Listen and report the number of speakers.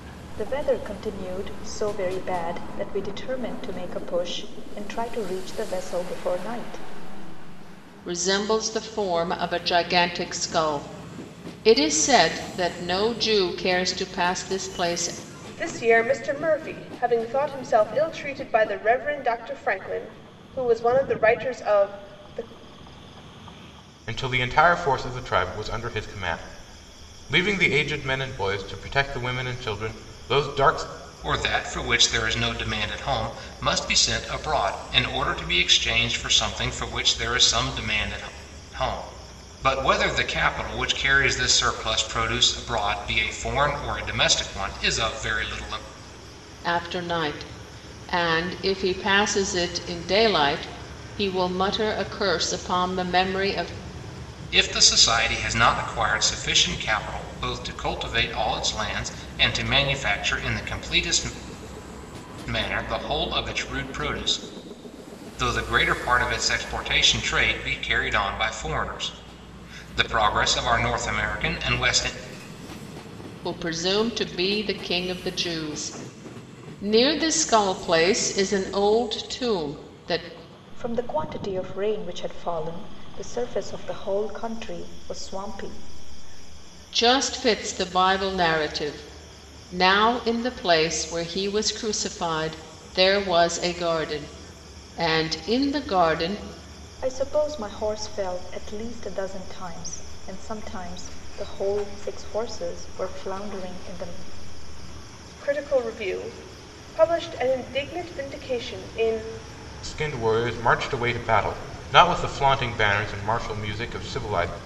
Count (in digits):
5